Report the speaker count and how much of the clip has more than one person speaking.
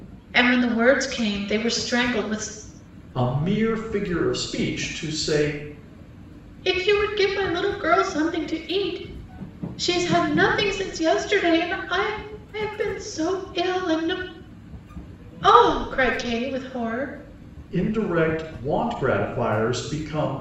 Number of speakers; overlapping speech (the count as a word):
two, no overlap